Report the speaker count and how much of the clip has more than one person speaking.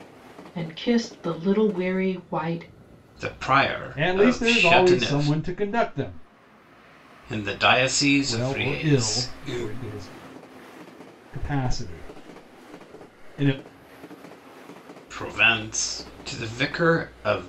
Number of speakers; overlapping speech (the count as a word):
three, about 16%